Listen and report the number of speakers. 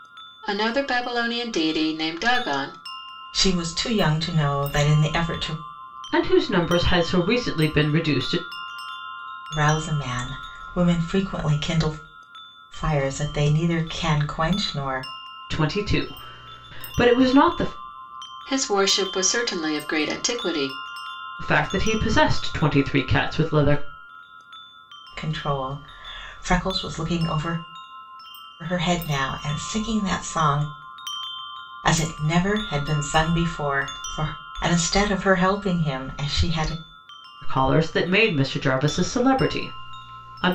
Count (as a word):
three